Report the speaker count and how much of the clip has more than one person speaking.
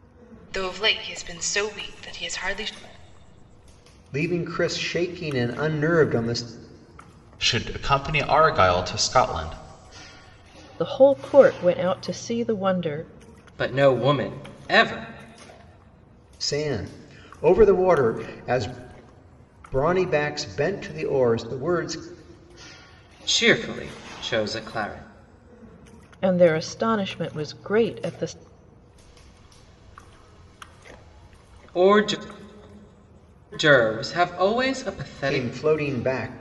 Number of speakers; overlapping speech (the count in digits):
5, about 1%